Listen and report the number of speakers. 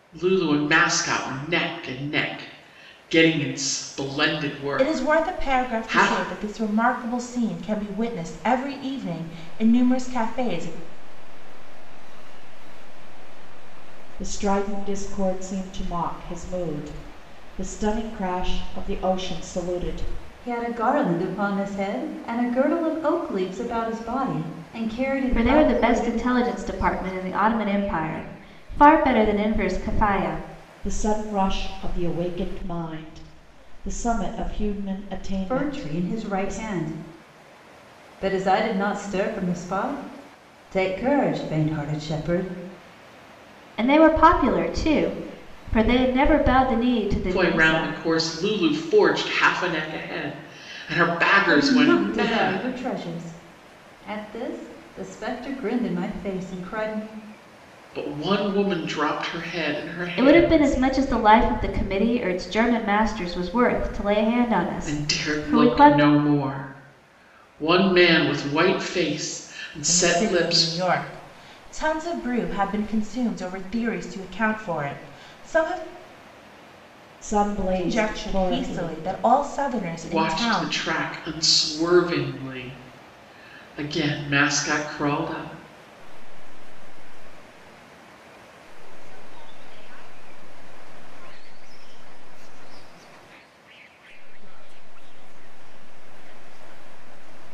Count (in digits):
6